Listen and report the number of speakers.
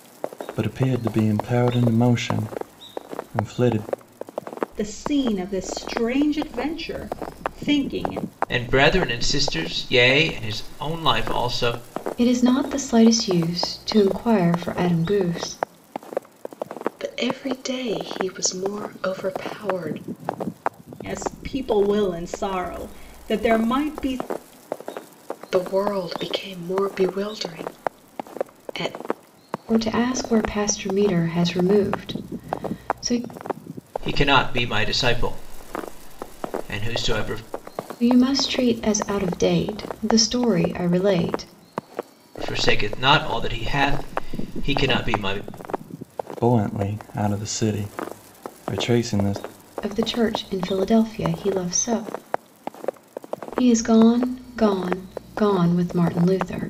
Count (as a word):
five